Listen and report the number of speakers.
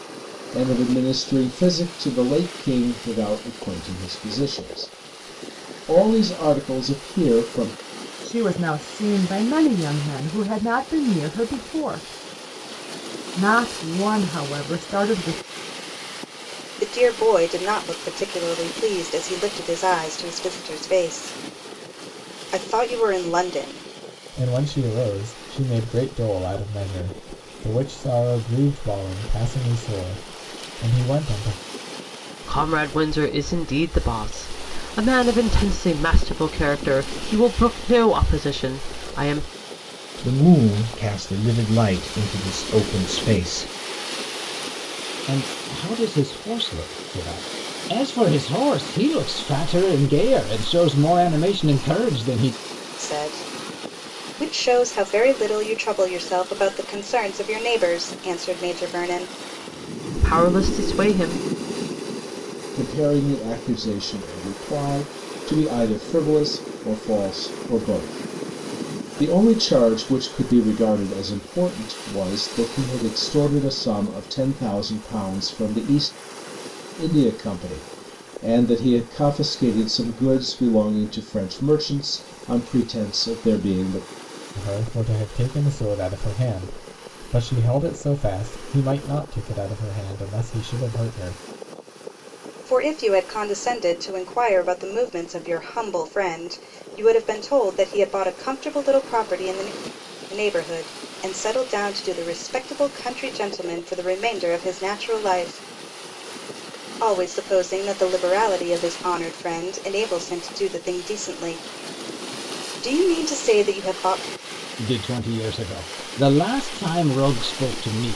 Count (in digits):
7